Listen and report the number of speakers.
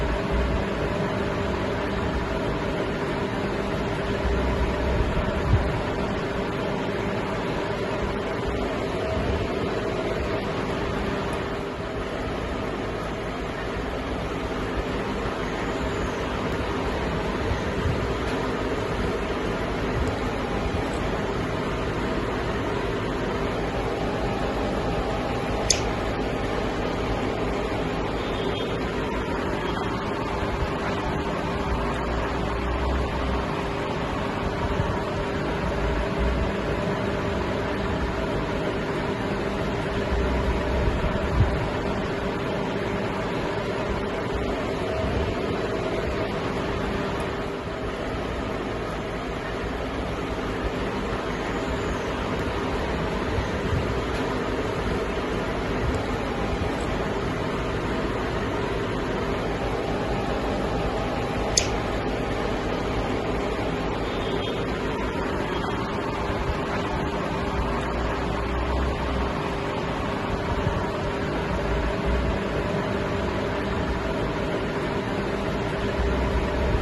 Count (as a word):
zero